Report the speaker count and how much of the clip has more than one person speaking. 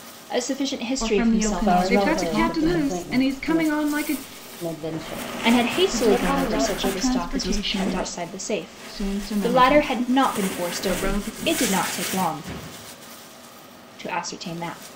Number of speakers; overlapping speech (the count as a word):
four, about 53%